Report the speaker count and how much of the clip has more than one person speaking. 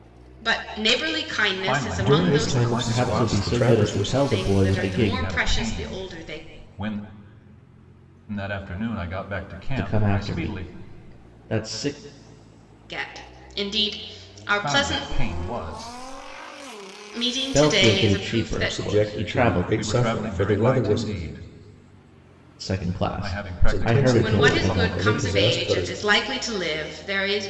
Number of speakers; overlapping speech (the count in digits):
4, about 47%